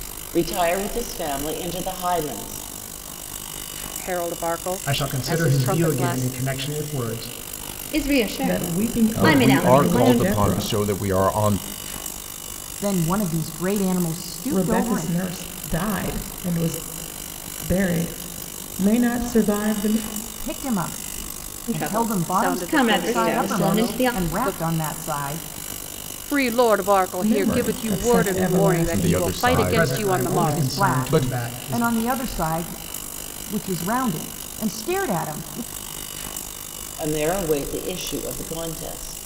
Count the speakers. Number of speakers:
seven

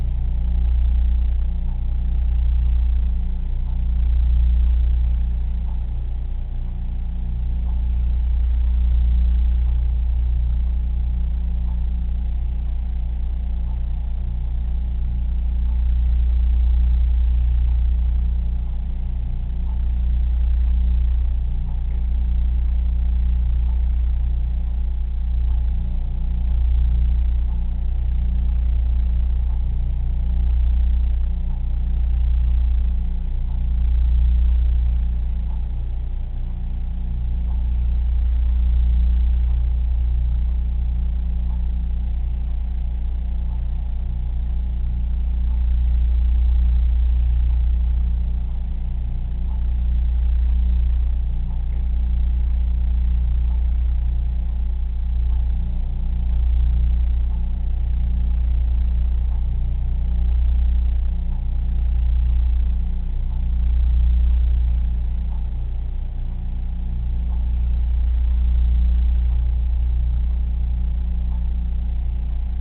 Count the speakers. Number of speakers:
zero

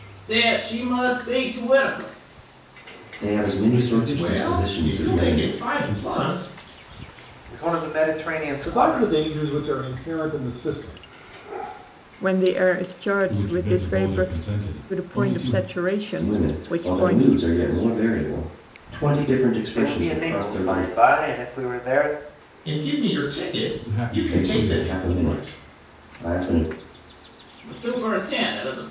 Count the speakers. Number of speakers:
seven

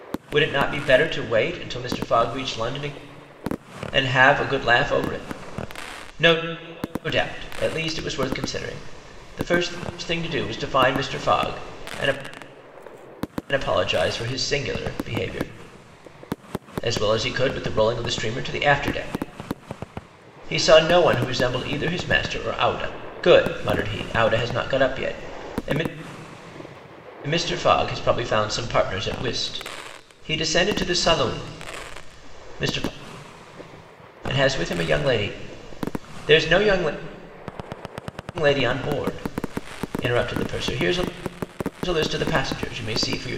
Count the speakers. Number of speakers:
one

